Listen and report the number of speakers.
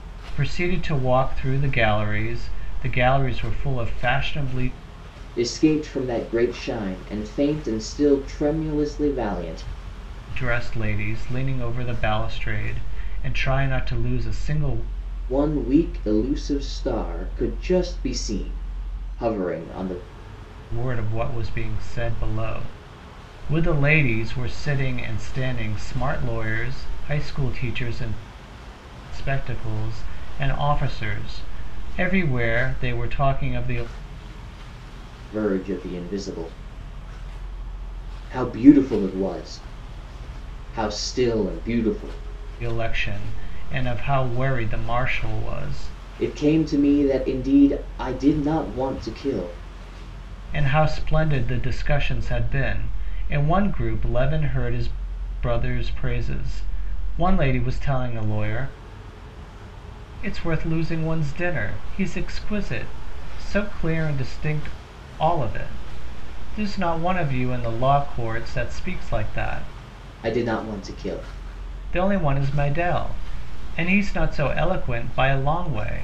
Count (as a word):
two